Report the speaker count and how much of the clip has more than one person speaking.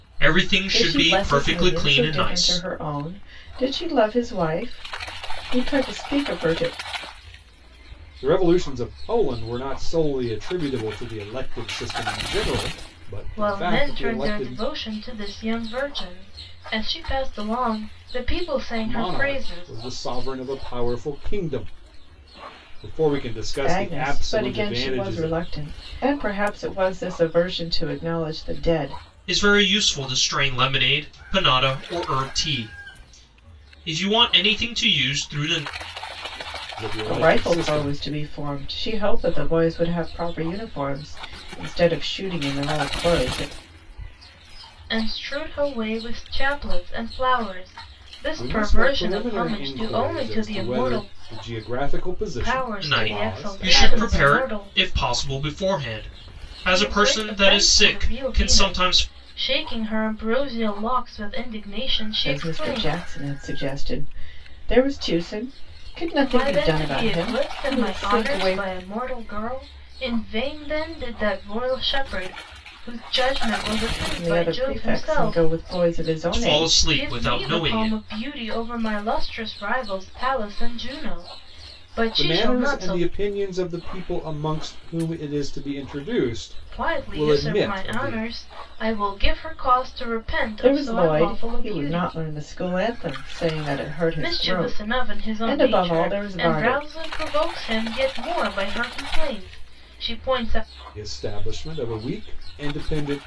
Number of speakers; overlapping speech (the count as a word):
four, about 27%